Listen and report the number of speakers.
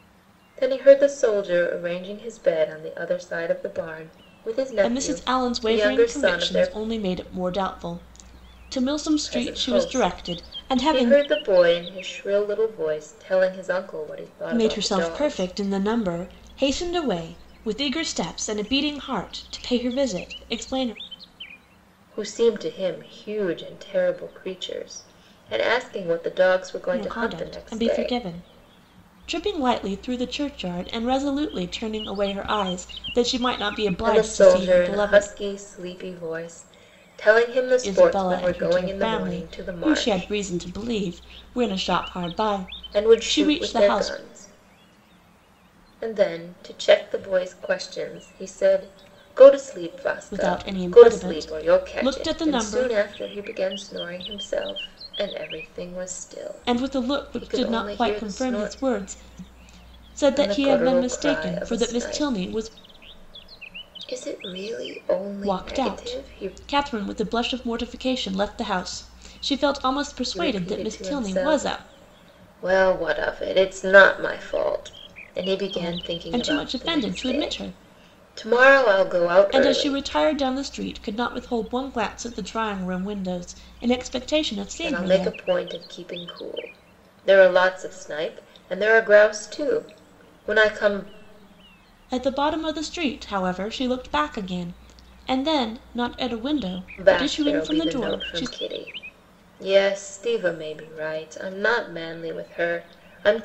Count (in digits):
2